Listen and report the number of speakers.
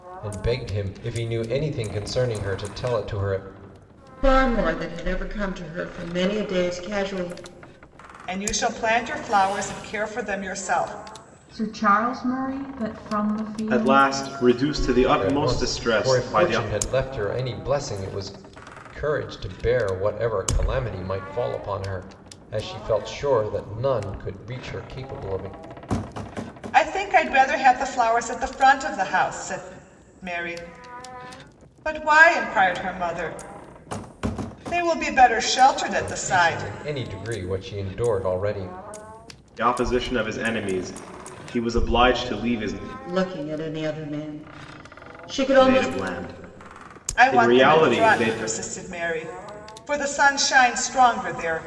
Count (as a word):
five